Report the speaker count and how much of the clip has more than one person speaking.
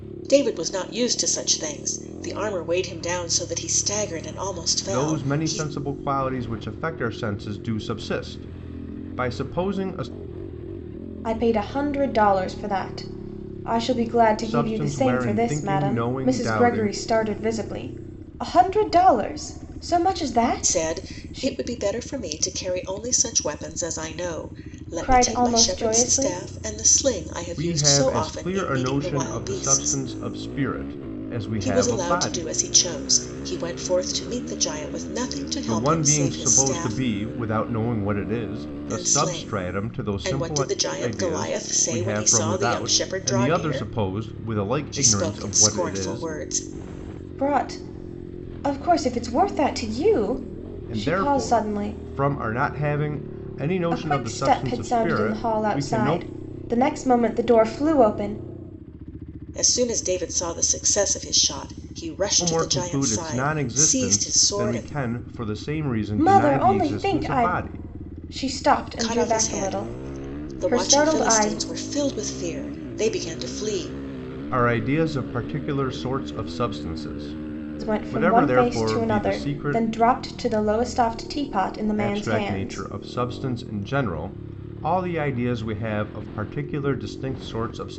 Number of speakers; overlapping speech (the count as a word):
three, about 34%